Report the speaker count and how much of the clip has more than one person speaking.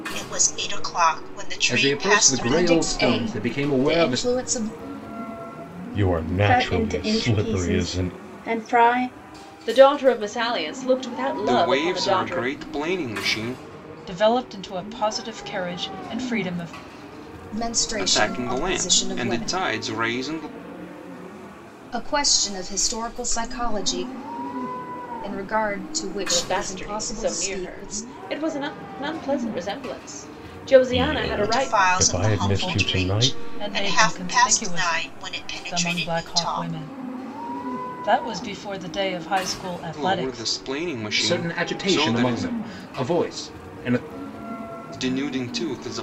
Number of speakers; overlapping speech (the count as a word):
eight, about 34%